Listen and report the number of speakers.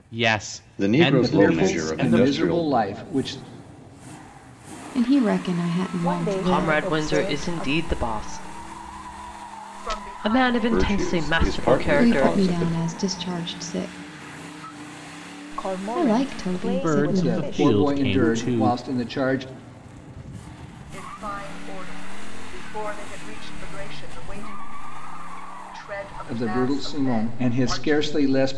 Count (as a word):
seven